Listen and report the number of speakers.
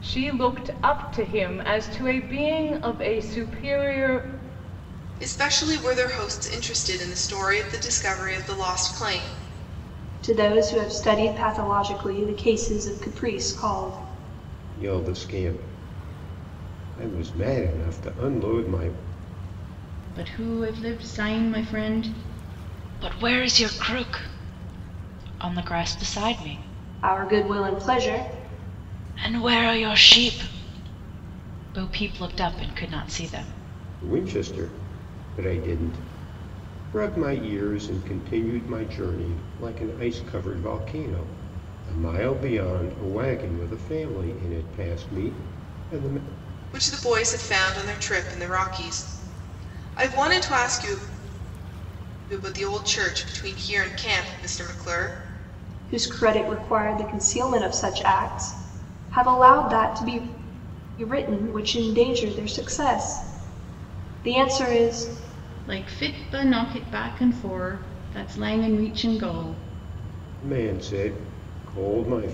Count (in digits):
6